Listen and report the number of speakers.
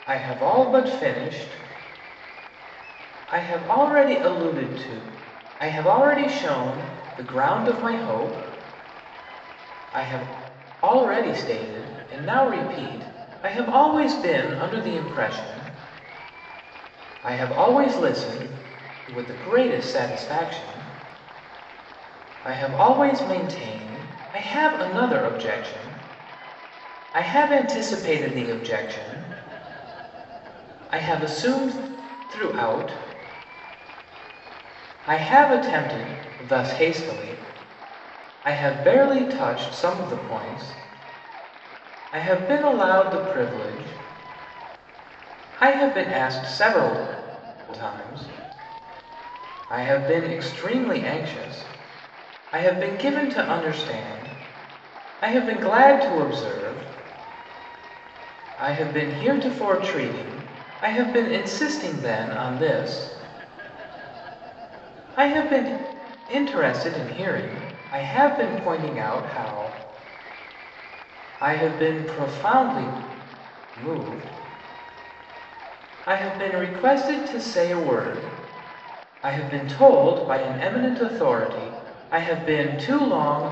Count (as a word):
one